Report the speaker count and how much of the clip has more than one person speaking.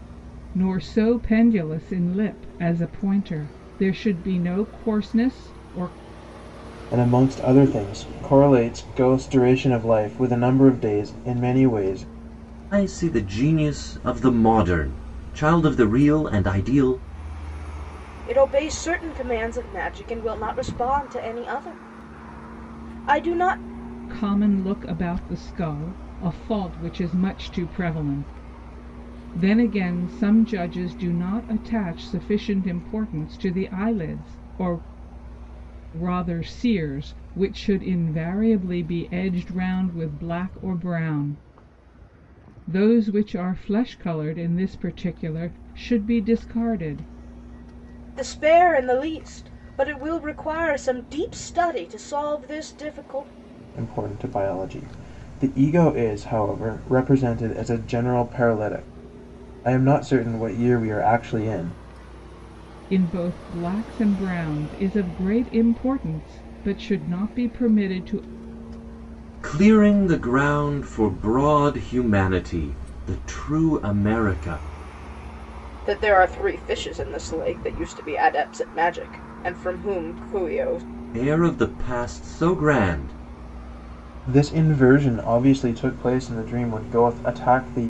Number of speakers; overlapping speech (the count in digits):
4, no overlap